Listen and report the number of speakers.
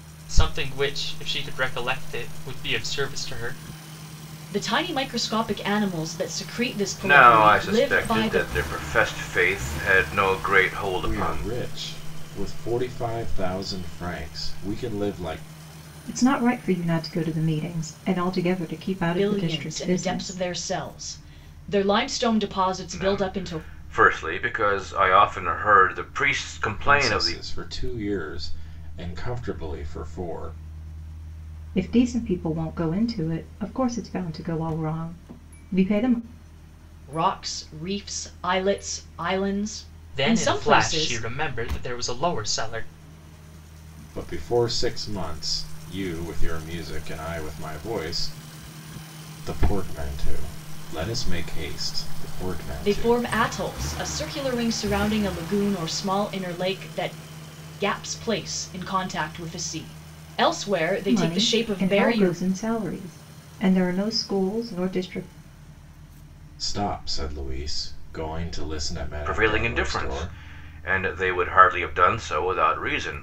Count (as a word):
five